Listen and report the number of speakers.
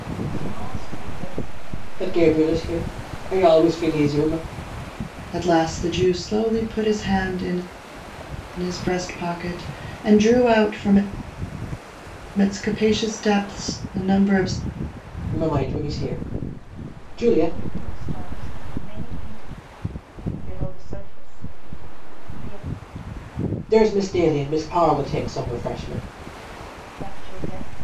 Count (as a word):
three